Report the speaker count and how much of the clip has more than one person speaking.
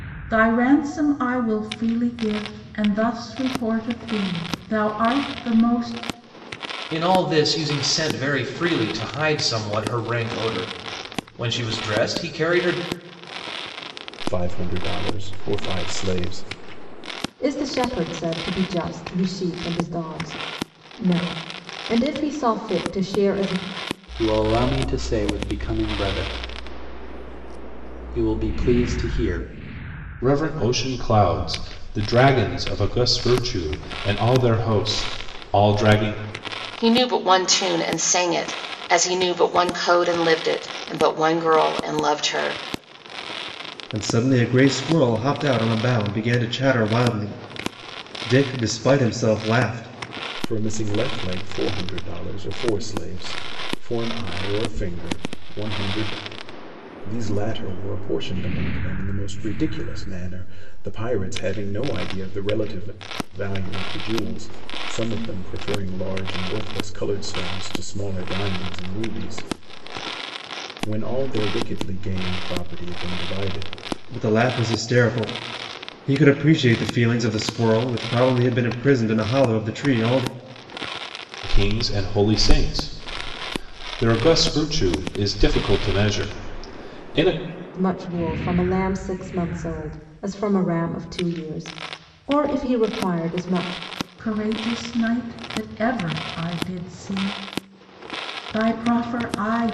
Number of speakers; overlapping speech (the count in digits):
8, no overlap